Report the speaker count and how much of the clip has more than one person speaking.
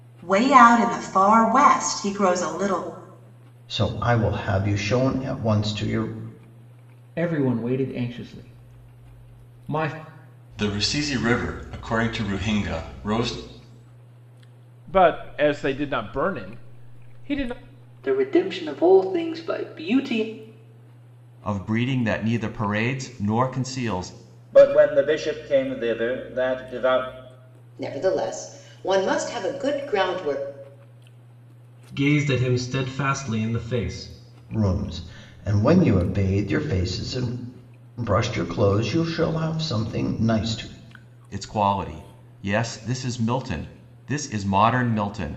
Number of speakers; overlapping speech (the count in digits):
10, no overlap